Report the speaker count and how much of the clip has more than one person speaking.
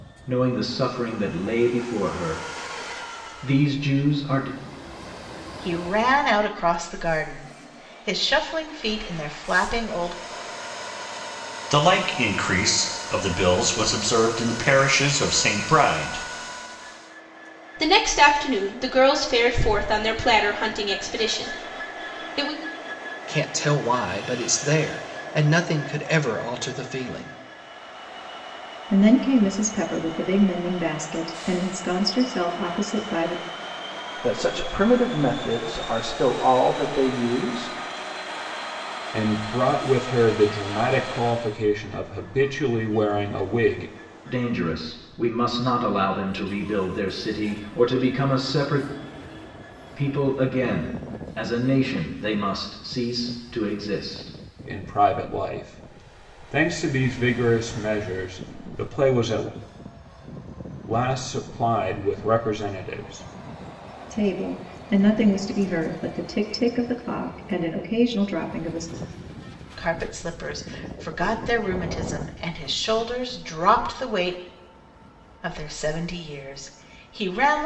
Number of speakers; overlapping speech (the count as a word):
eight, no overlap